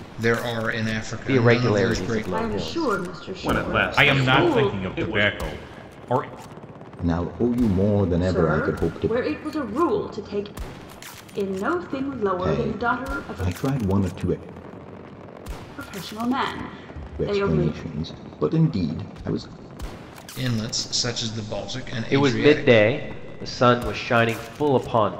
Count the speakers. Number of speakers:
six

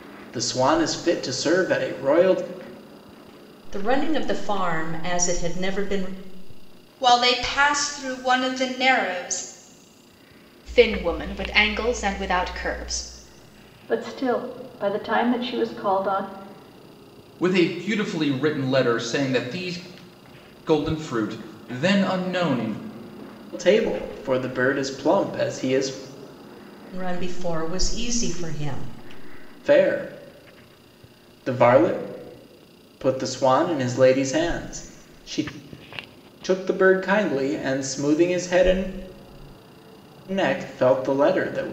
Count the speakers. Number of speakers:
six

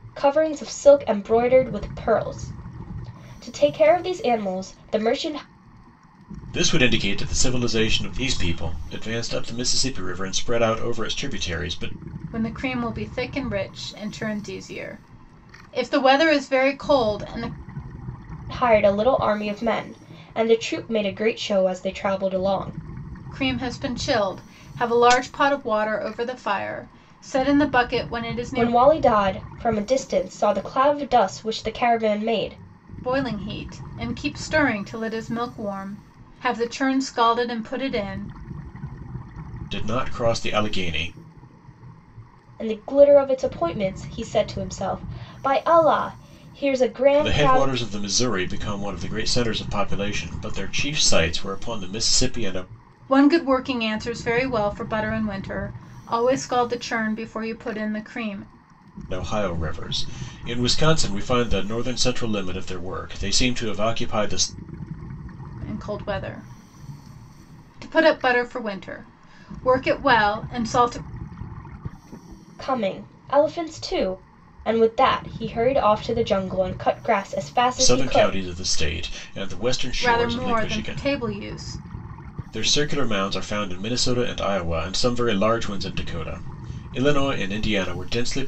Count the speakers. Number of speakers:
three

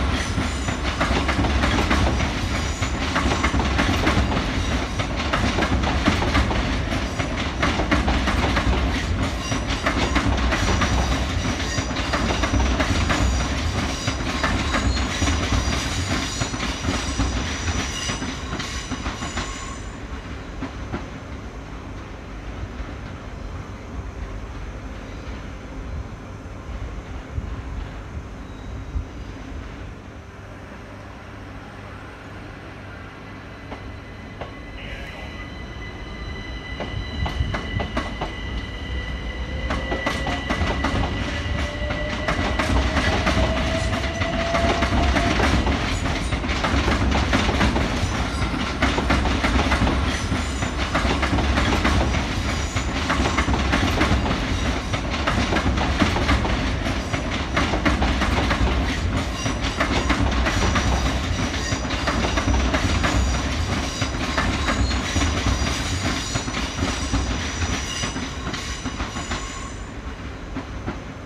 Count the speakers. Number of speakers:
zero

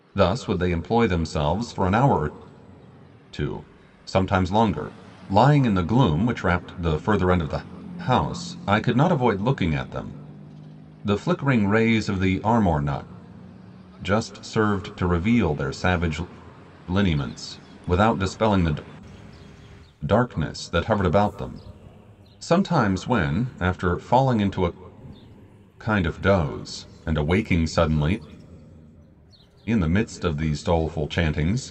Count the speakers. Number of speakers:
one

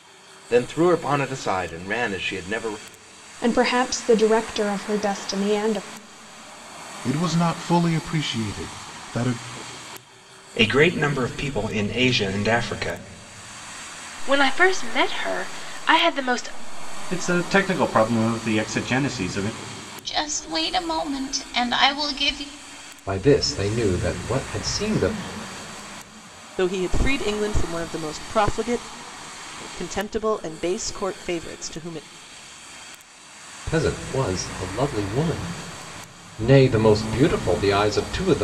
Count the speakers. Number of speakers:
nine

